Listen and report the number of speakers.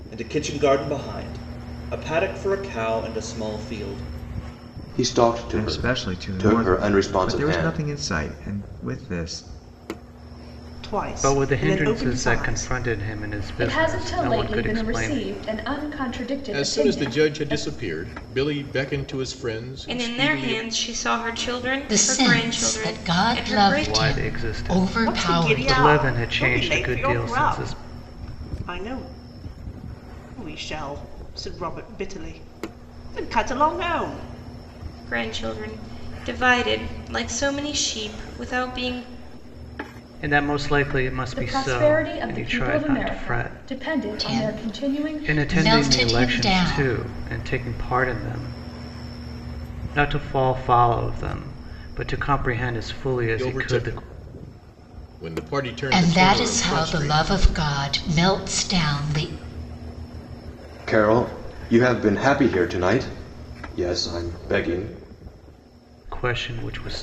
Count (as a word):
nine